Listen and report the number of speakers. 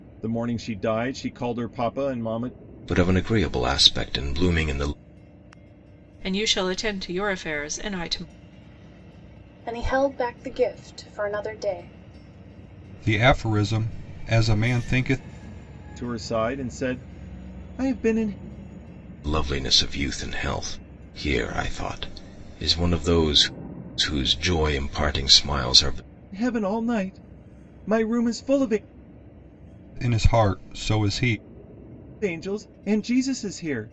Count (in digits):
5